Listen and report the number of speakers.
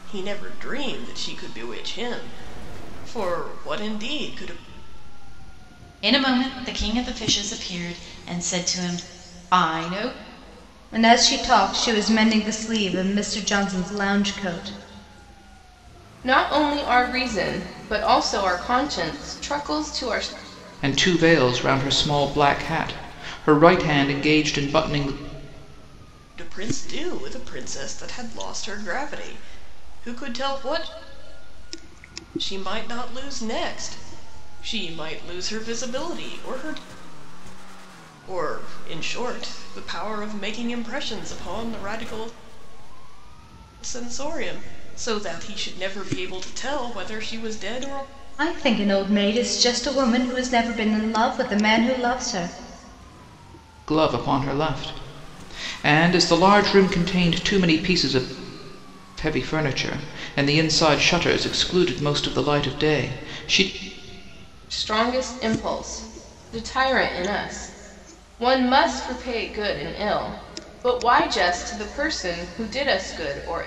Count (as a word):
five